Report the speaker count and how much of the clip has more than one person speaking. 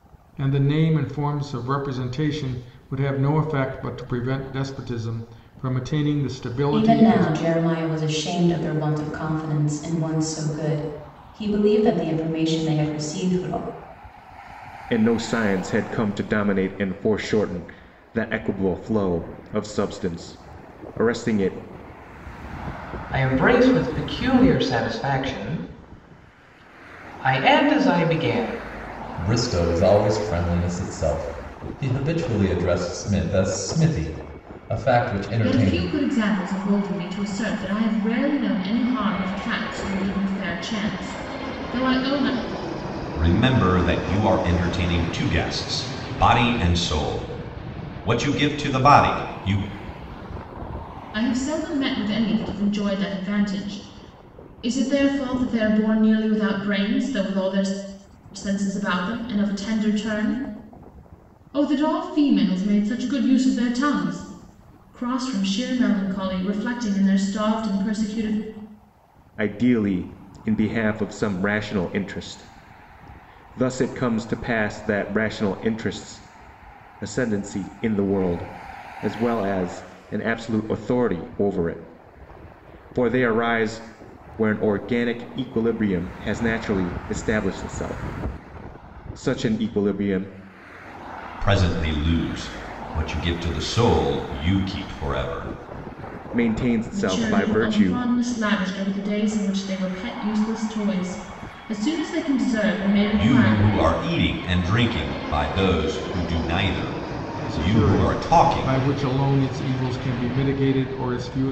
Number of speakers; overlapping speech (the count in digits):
7, about 4%